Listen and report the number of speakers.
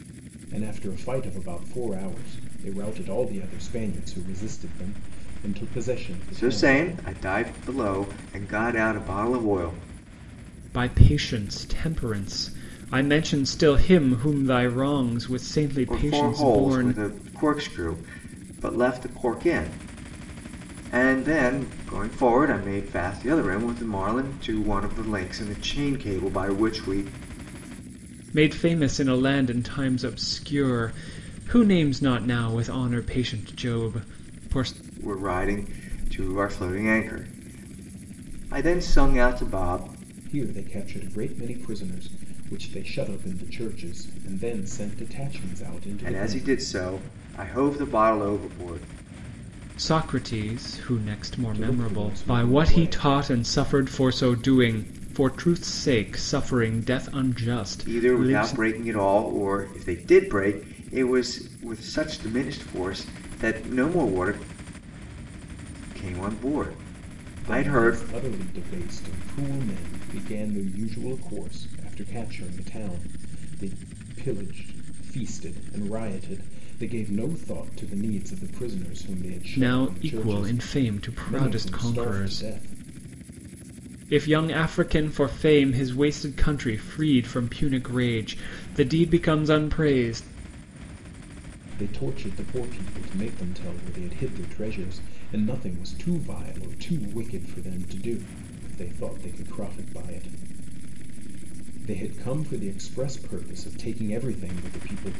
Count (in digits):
3